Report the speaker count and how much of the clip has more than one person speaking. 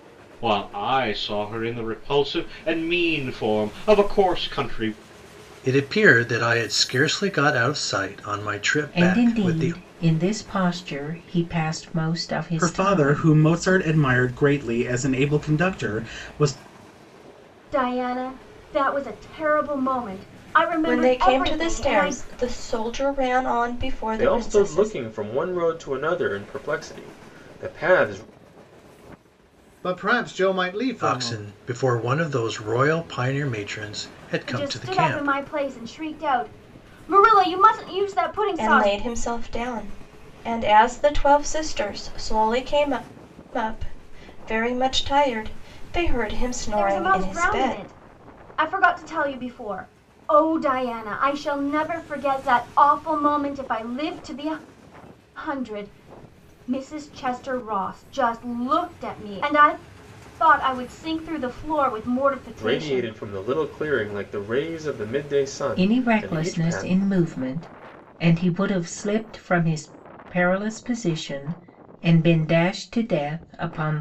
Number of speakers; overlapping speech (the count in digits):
8, about 12%